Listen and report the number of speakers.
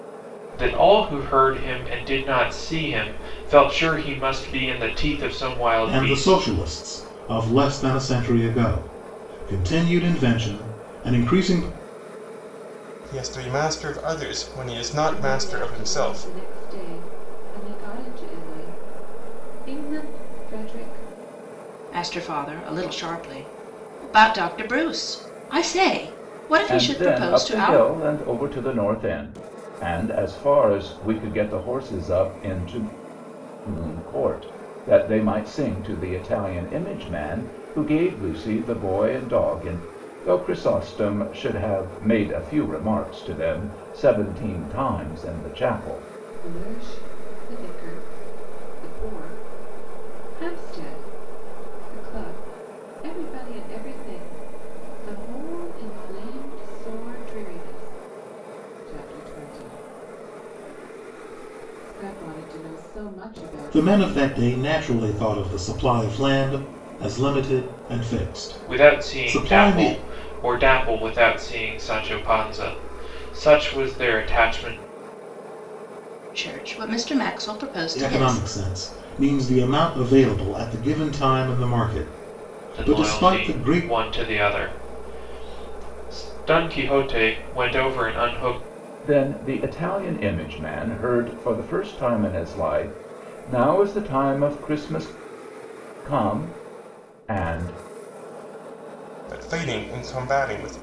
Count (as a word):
six